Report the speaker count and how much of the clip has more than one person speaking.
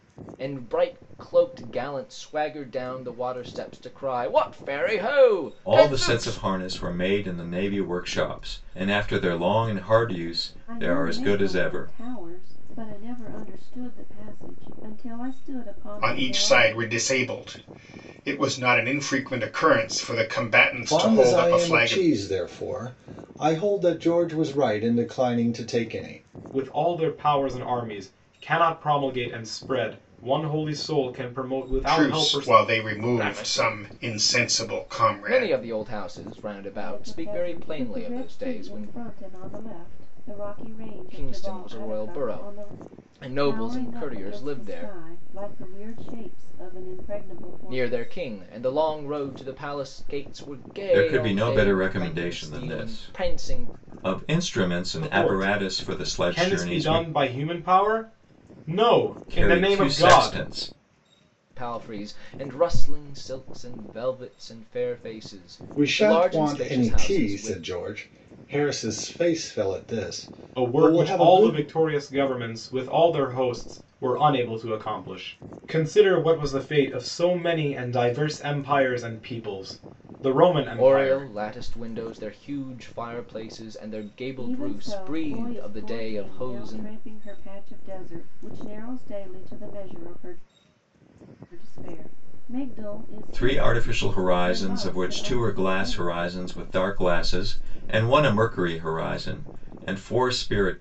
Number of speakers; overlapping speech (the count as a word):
six, about 28%